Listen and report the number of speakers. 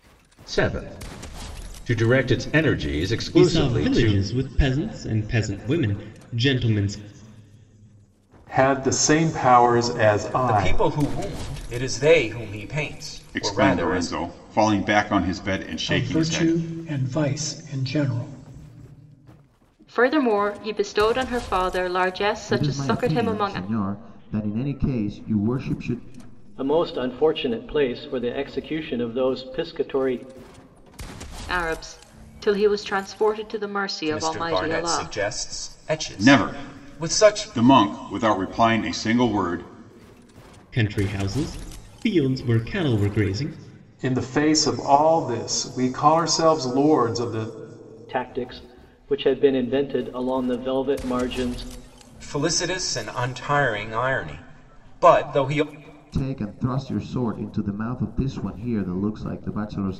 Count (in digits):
9